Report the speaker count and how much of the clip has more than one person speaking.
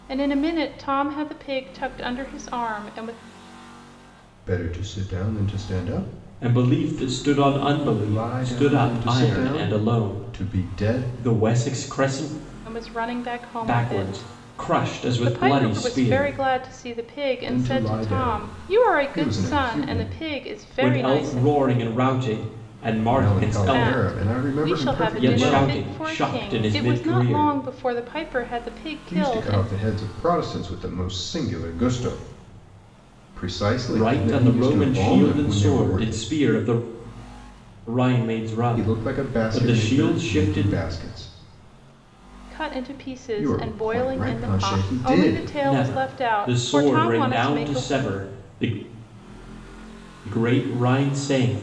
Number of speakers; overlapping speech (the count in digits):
3, about 46%